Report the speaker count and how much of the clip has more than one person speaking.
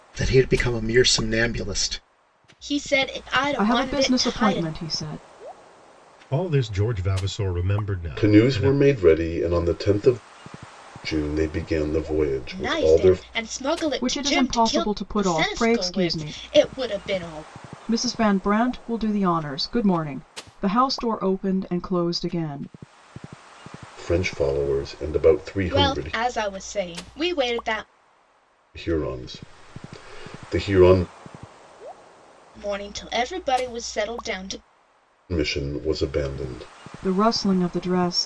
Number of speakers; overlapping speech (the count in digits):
5, about 14%